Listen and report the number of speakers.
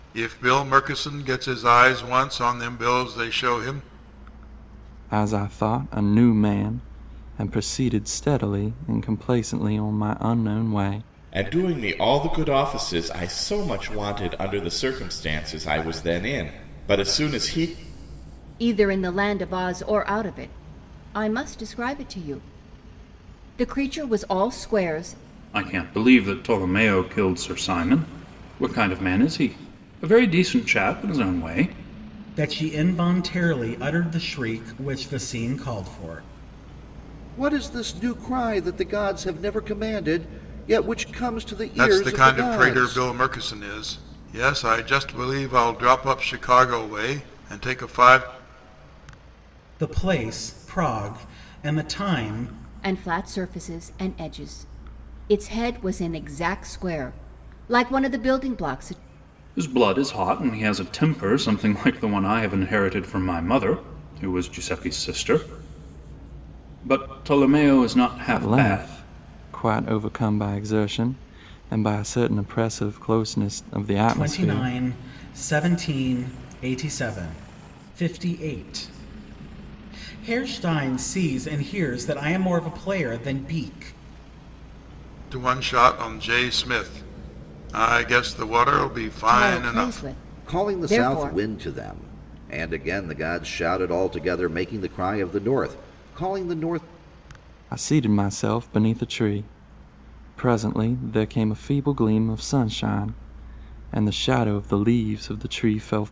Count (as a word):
seven